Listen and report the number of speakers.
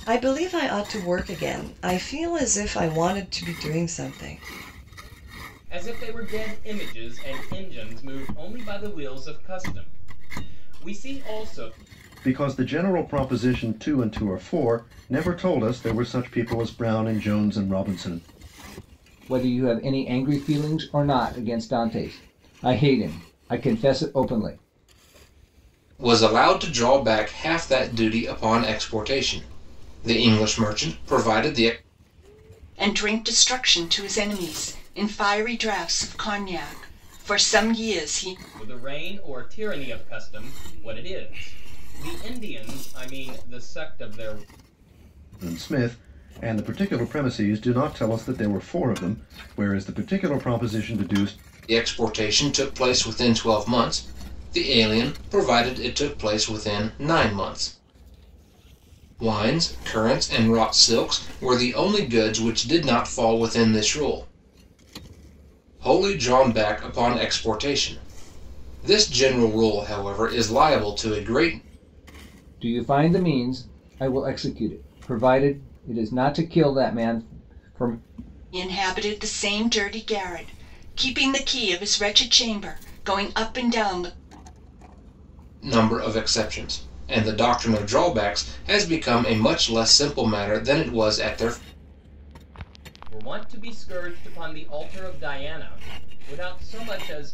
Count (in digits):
6